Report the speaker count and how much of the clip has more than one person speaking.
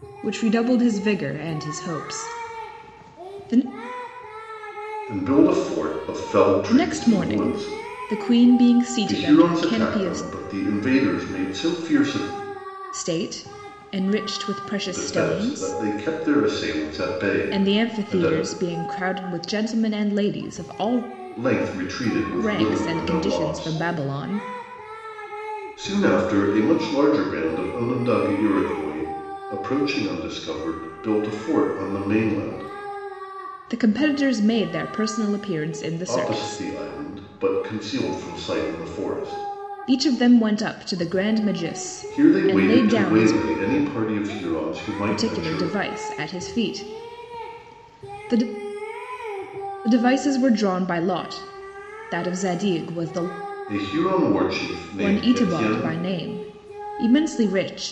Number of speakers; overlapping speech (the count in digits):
2, about 16%